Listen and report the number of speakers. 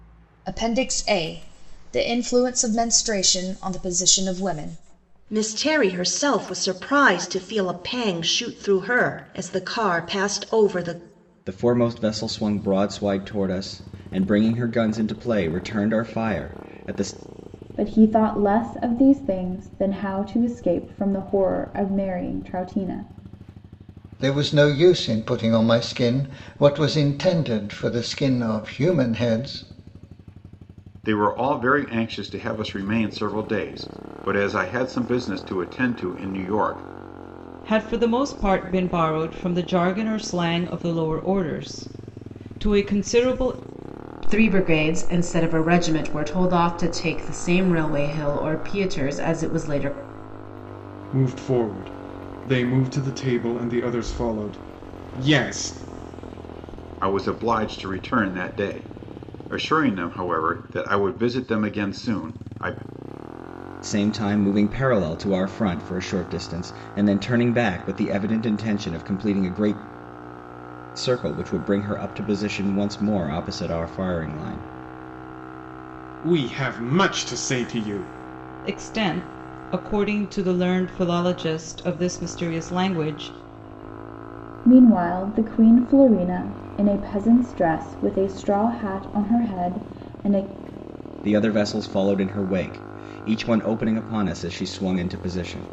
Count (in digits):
9